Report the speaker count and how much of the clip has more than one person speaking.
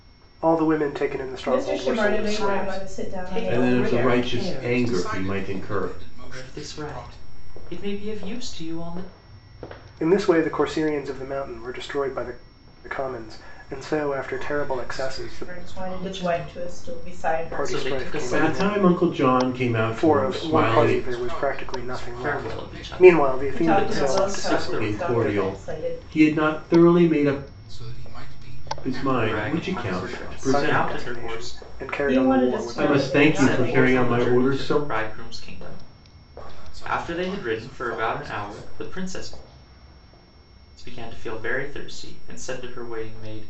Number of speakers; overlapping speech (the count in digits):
5, about 54%